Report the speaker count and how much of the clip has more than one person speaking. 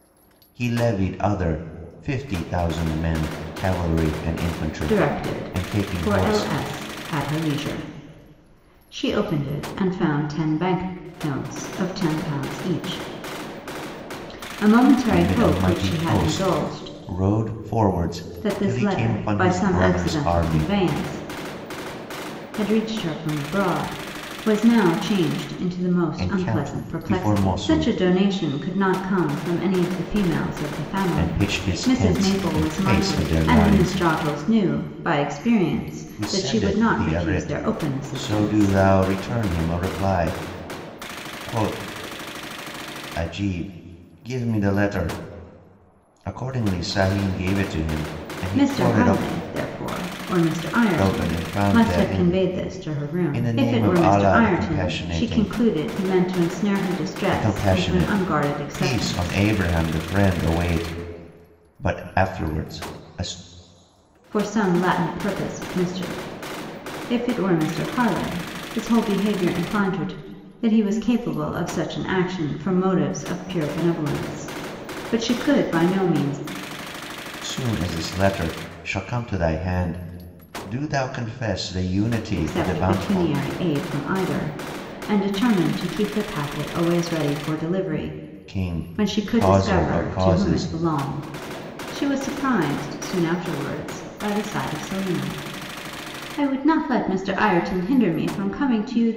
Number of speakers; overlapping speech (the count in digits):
2, about 24%